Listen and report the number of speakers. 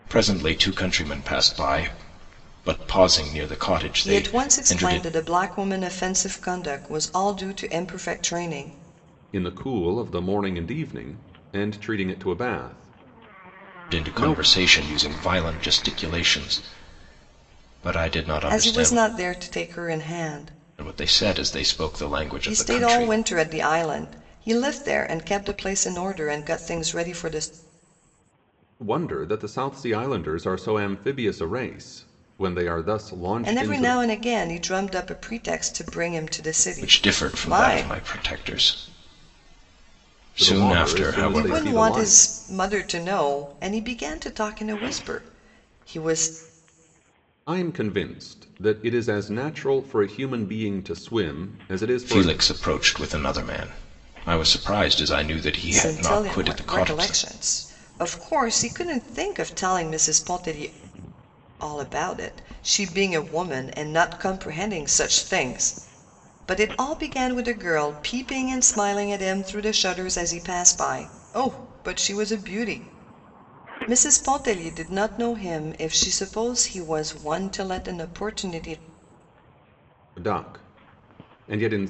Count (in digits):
3